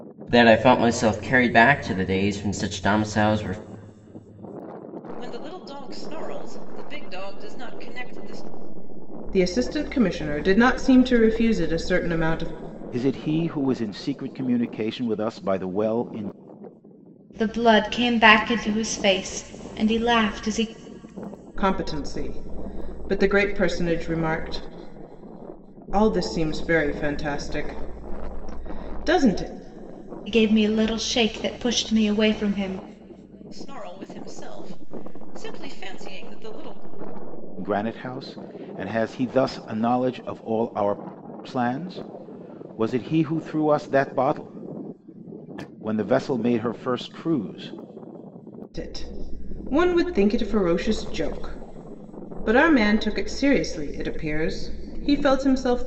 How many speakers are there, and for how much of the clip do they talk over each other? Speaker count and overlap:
five, no overlap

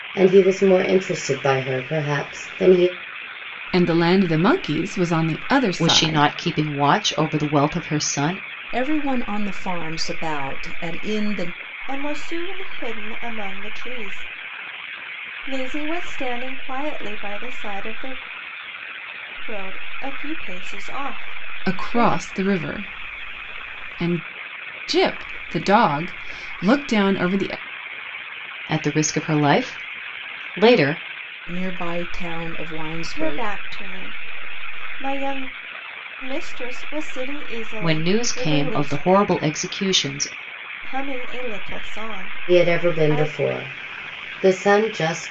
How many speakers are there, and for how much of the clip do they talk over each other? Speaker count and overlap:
five, about 8%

